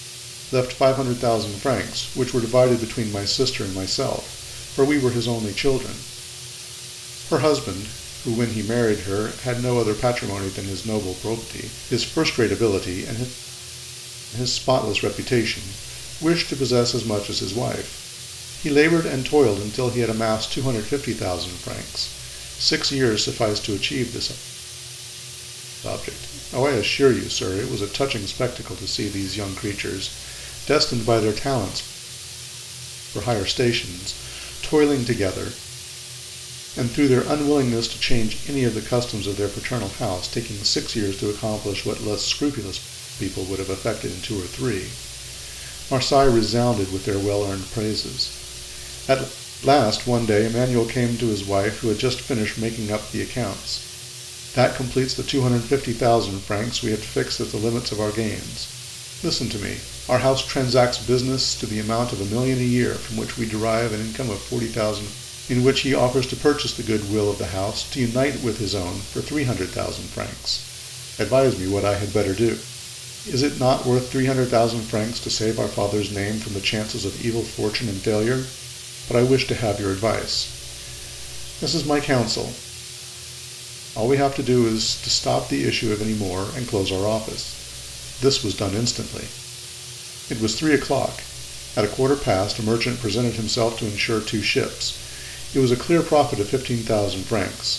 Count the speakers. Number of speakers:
one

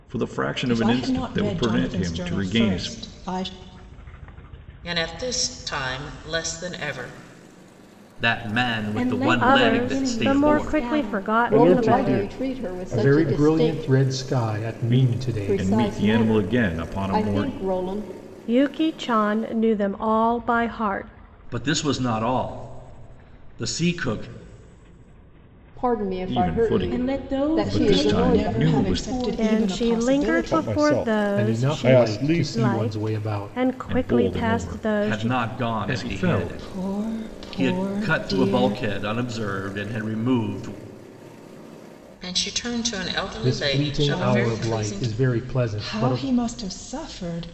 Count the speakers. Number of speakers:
nine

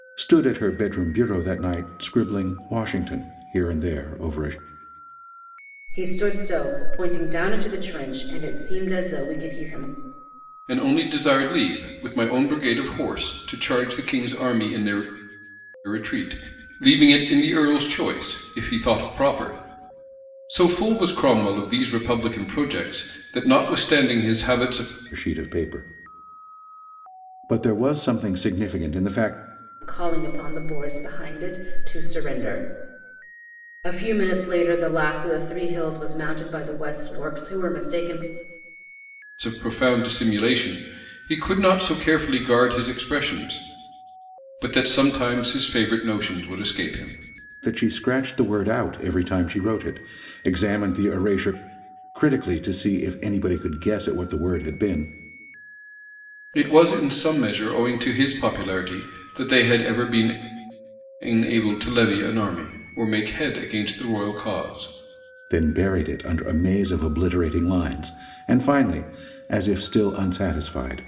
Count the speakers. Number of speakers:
three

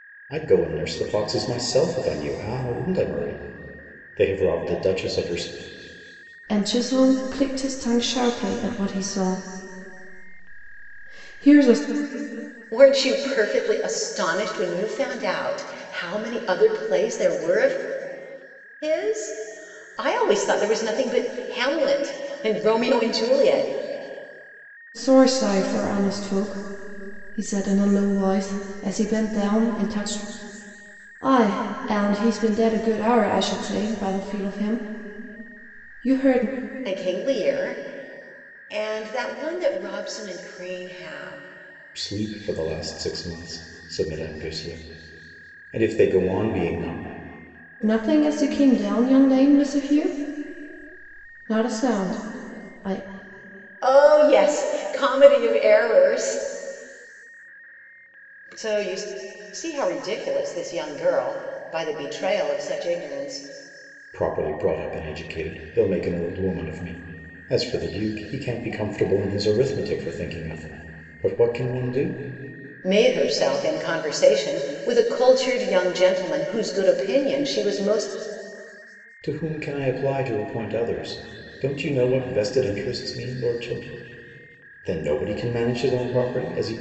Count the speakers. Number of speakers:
three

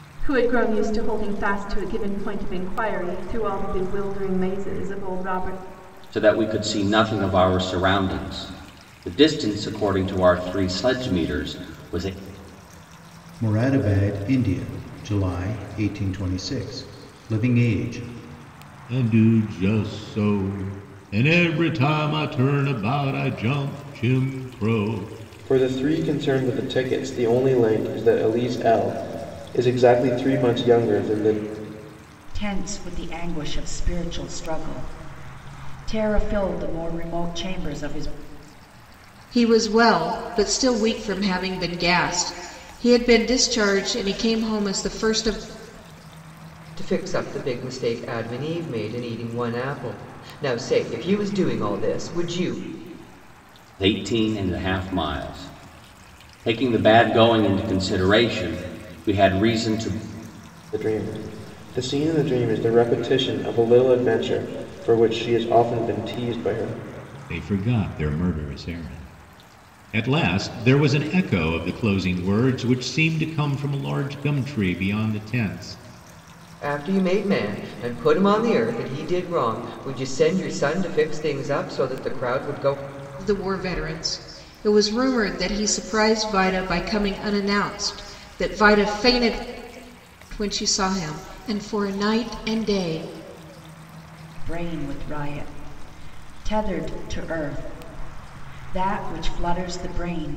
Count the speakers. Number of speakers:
eight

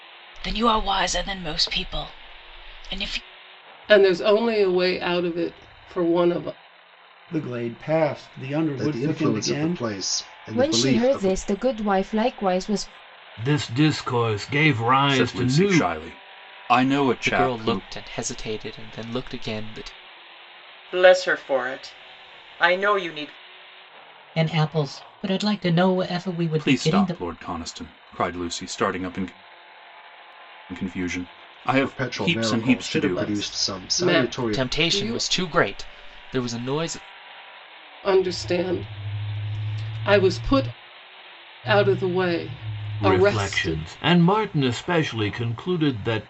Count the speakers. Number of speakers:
ten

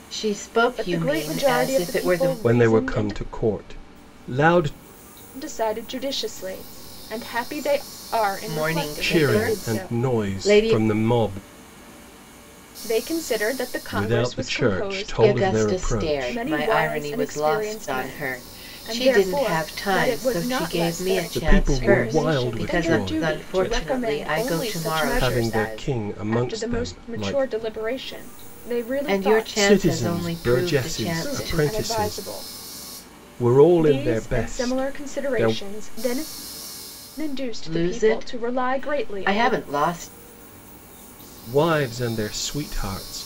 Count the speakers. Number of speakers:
three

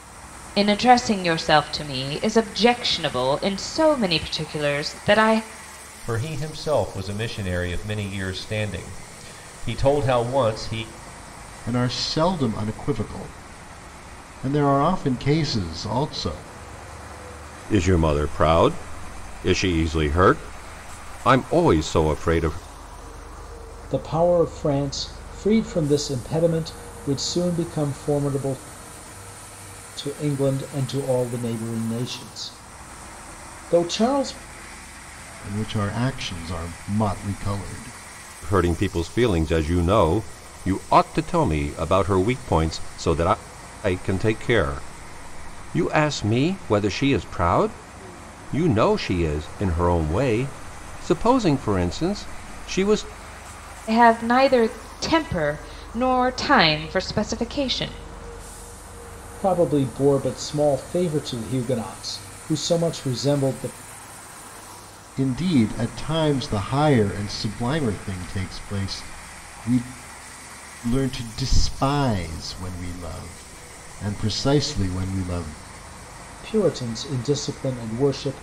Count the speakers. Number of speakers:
five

